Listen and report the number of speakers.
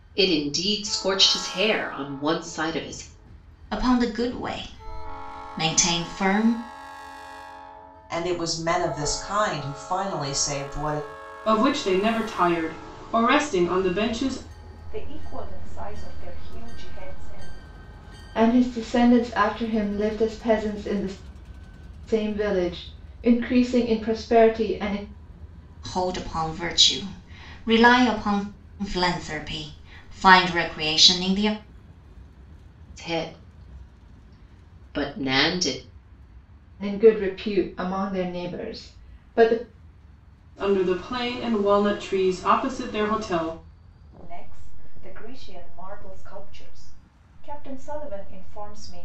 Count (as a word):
six